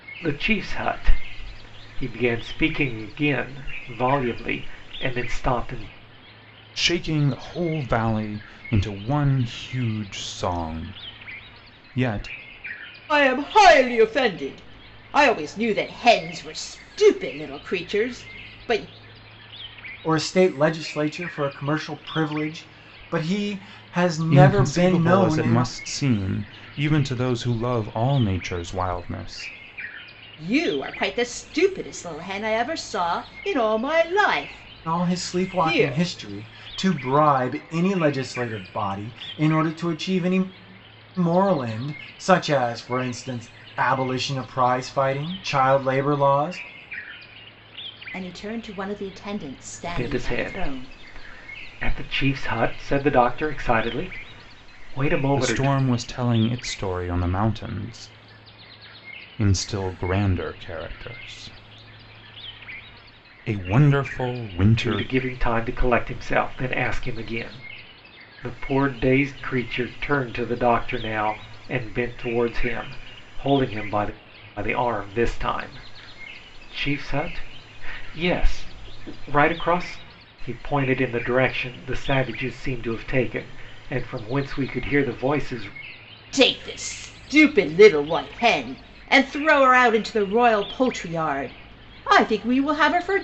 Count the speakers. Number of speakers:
4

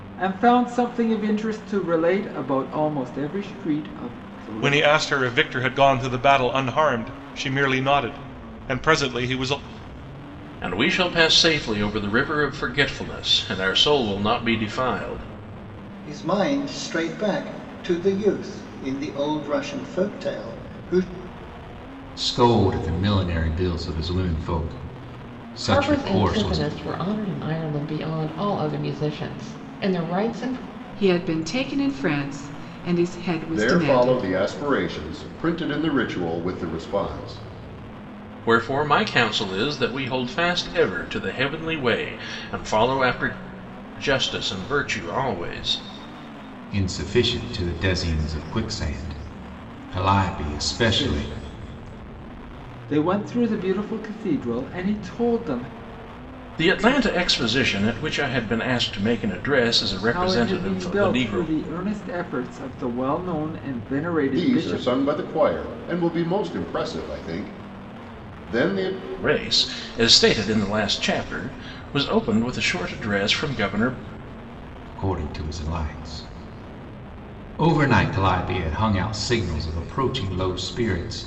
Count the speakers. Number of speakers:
8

